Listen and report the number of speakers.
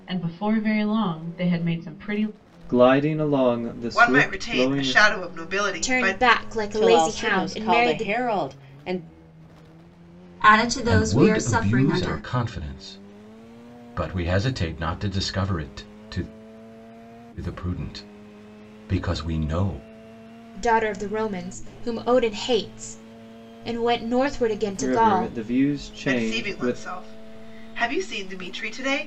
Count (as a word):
seven